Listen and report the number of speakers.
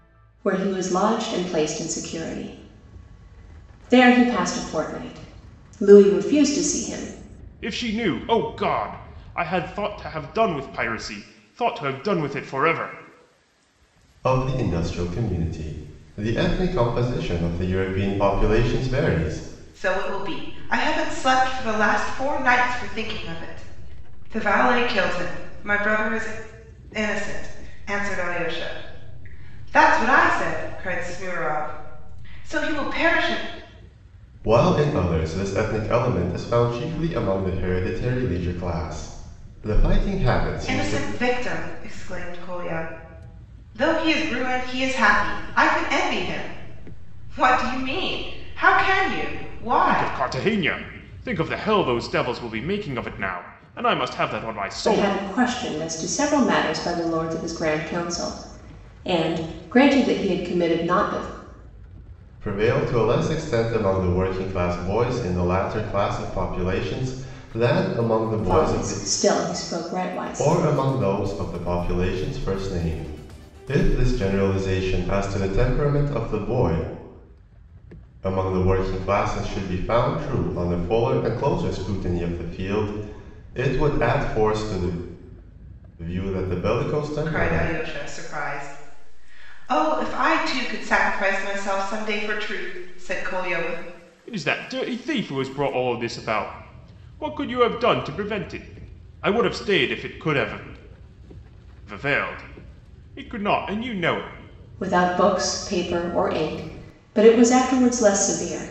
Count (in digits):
4